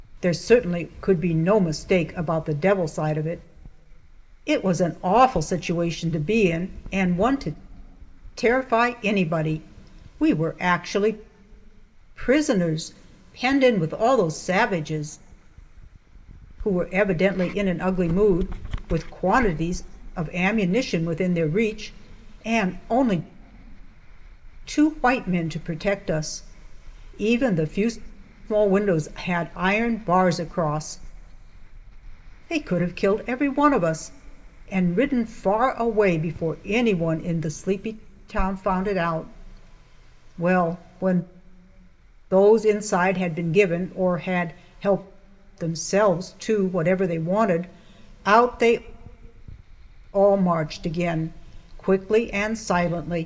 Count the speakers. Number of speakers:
1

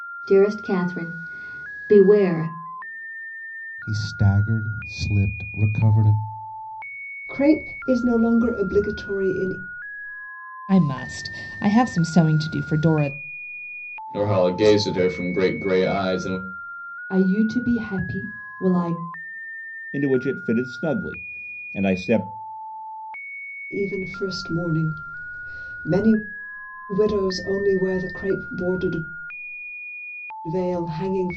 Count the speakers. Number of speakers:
7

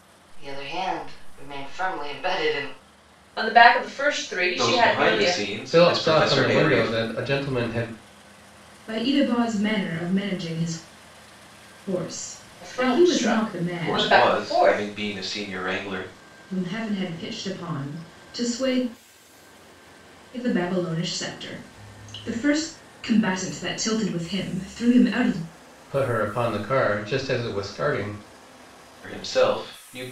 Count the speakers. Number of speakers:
5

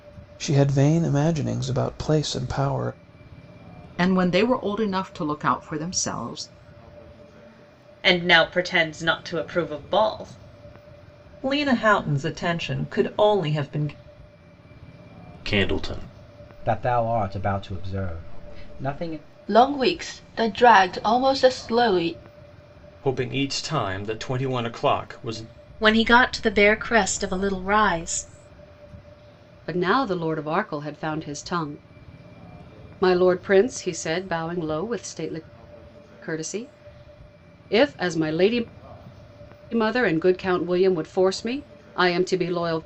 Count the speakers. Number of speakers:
10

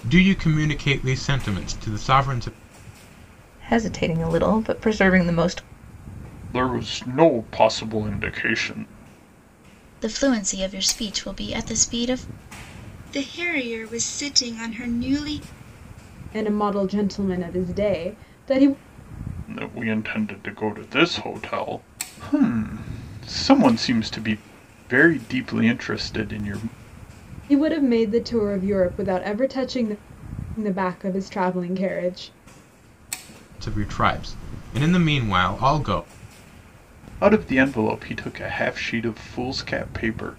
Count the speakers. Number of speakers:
6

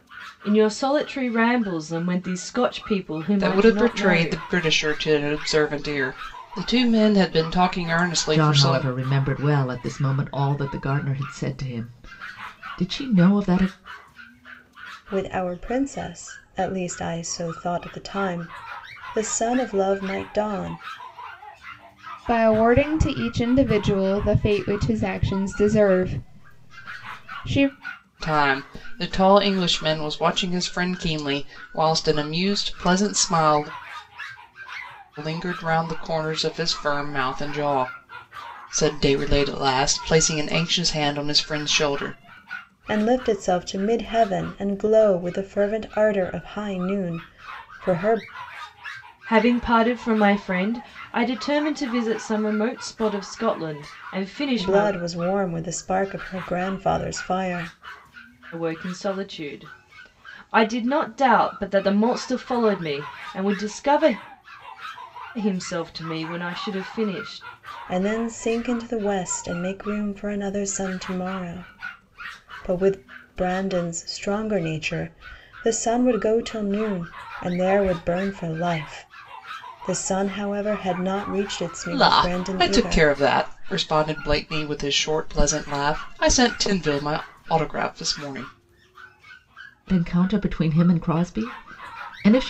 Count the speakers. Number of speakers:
5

